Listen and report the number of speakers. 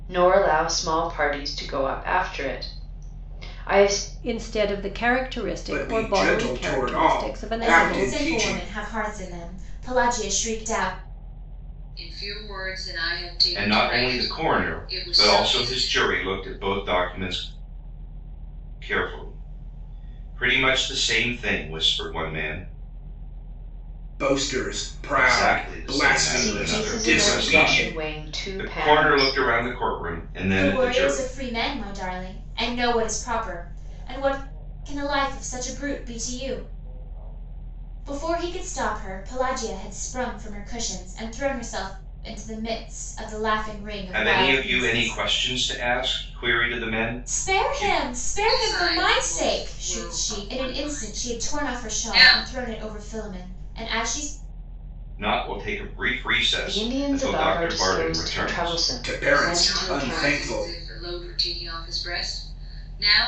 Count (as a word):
six